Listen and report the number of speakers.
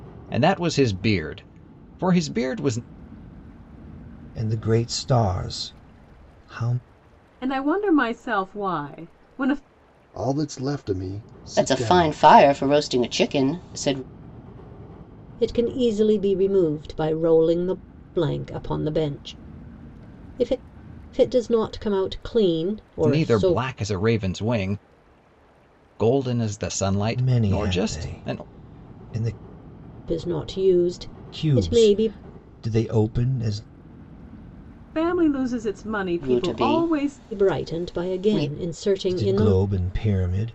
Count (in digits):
6